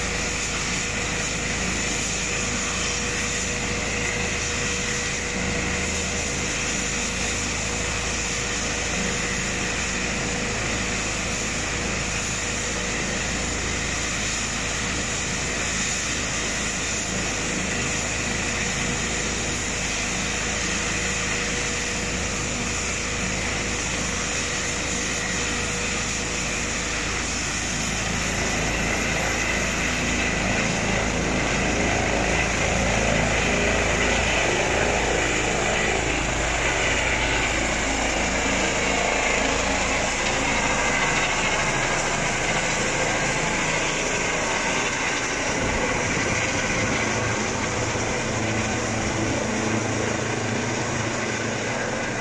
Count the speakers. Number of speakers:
0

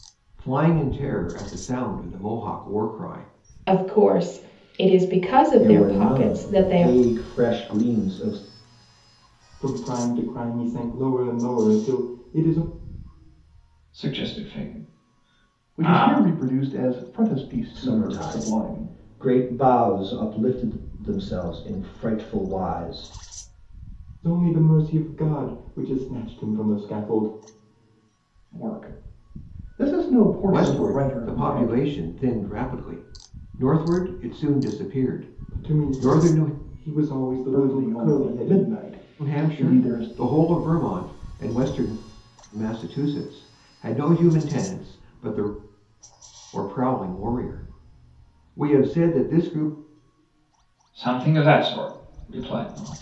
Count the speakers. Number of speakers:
6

